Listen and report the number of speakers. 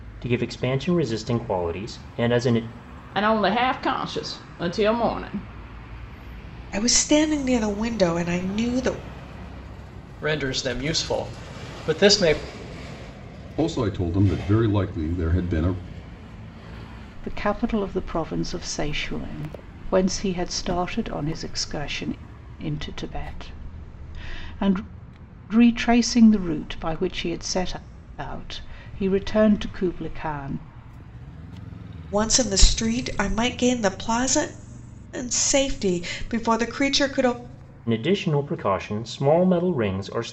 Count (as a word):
six